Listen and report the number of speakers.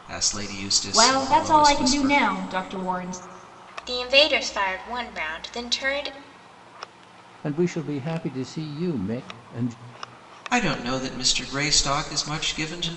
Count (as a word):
four